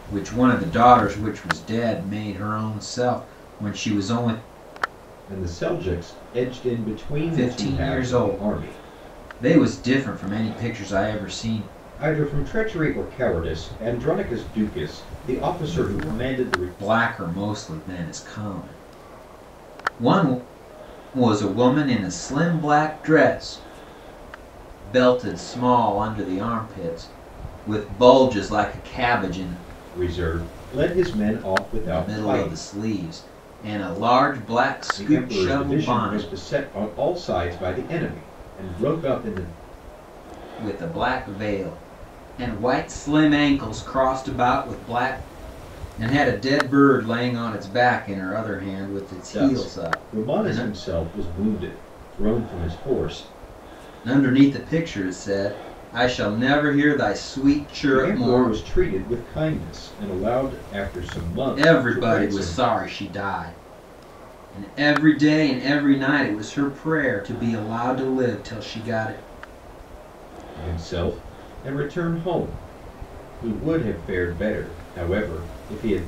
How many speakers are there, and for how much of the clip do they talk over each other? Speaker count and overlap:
2, about 10%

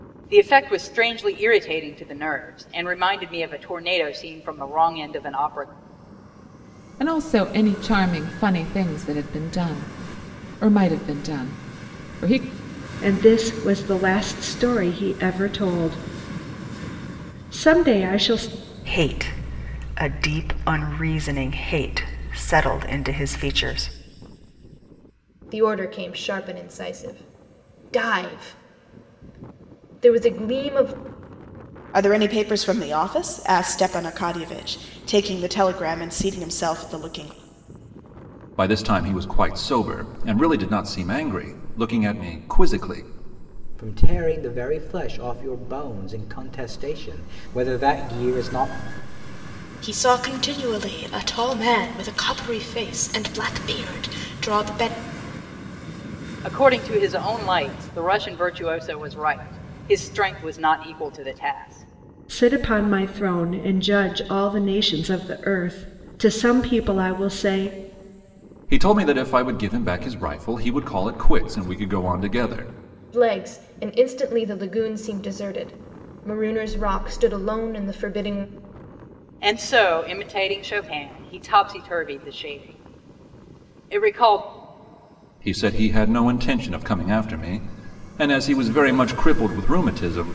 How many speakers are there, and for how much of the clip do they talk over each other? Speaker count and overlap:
9, no overlap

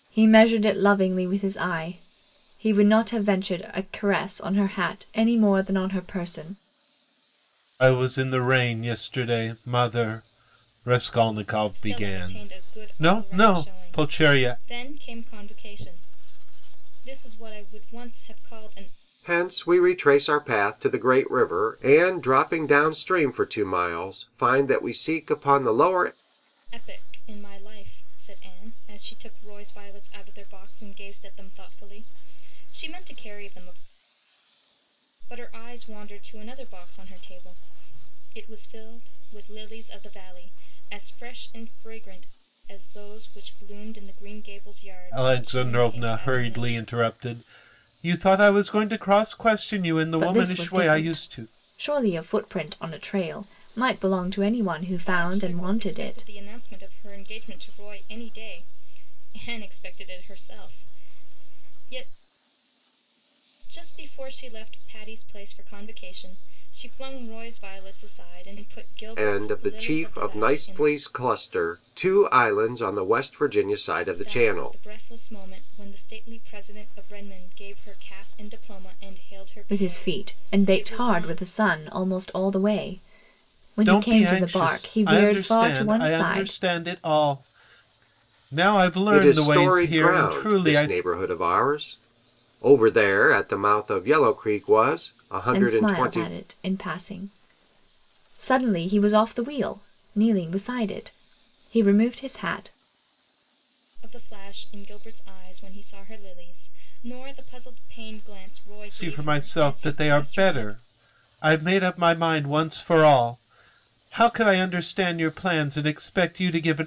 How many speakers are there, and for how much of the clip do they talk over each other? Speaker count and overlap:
4, about 16%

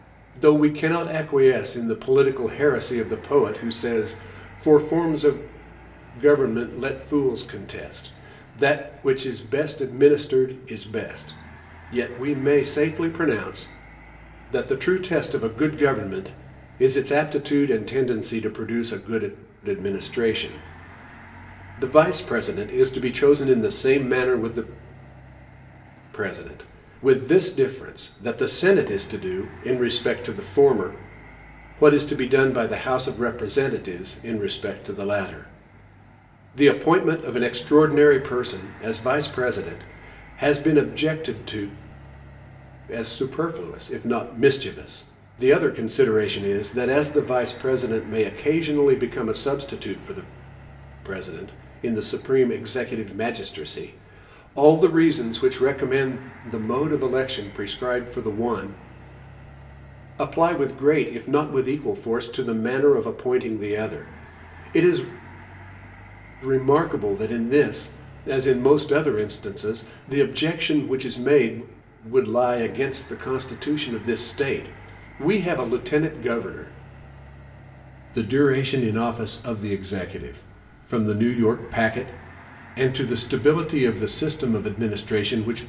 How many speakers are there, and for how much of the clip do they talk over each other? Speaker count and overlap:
1, no overlap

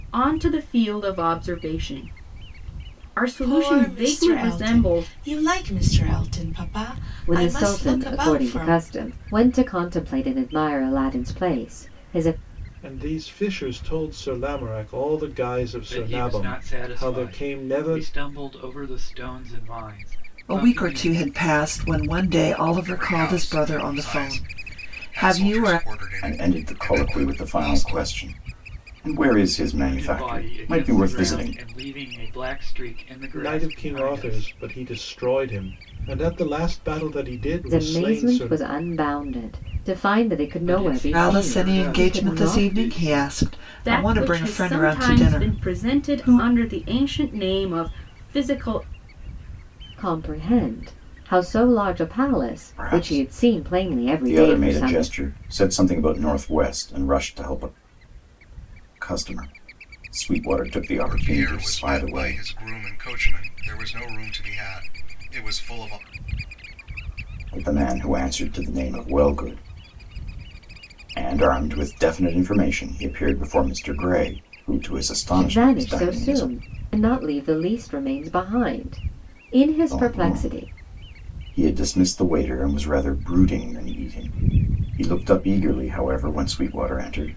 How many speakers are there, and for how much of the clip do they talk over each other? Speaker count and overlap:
8, about 30%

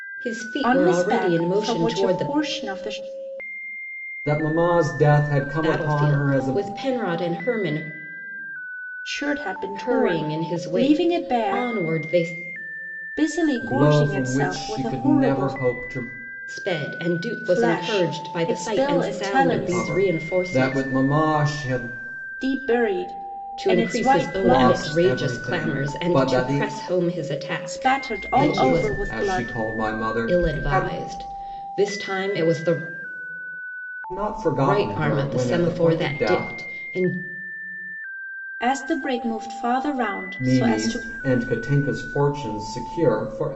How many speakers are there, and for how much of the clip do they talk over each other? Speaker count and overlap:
3, about 43%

